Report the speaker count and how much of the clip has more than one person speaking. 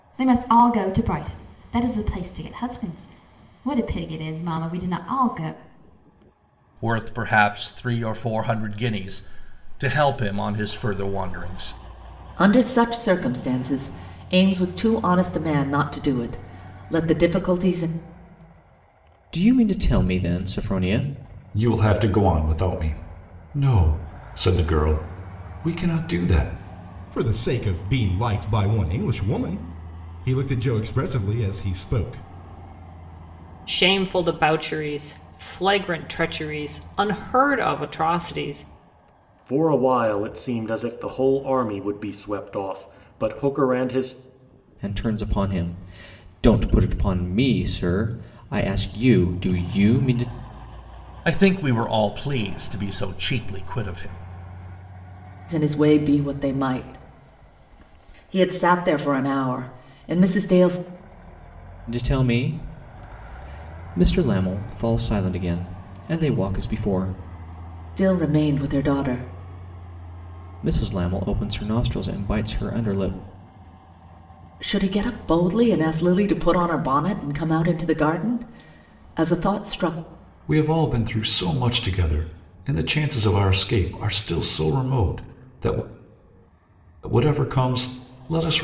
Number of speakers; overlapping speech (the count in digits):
8, no overlap